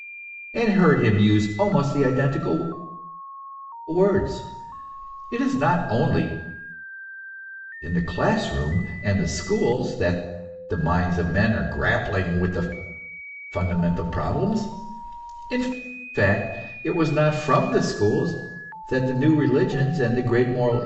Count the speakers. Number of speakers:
one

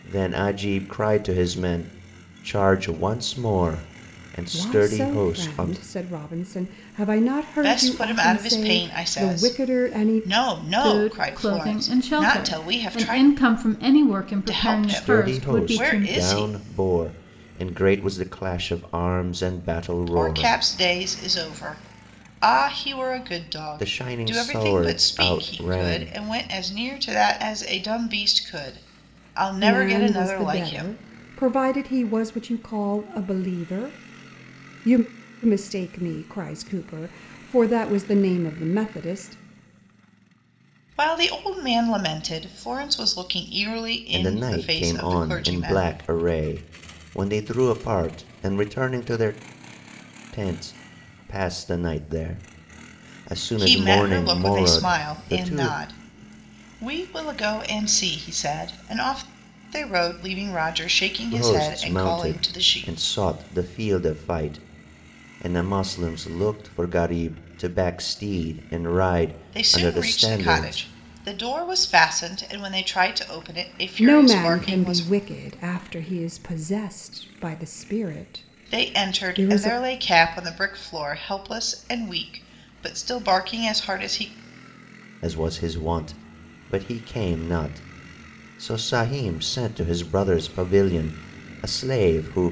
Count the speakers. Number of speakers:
four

